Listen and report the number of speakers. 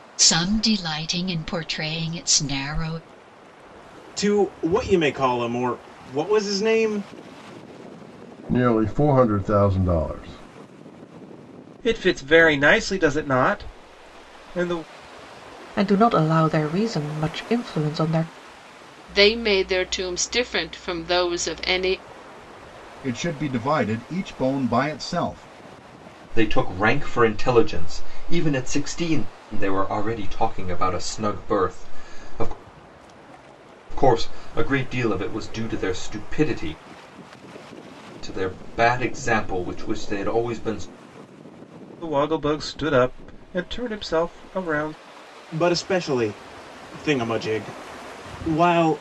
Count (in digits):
8